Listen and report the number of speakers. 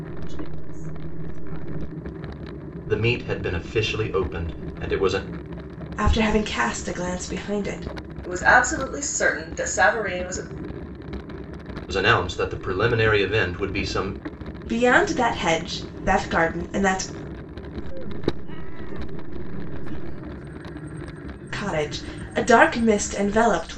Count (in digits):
4